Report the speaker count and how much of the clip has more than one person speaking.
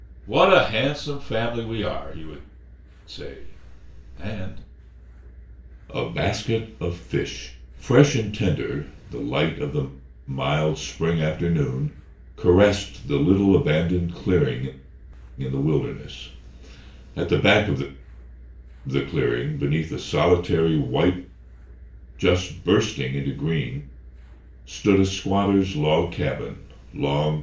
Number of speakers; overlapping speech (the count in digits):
1, no overlap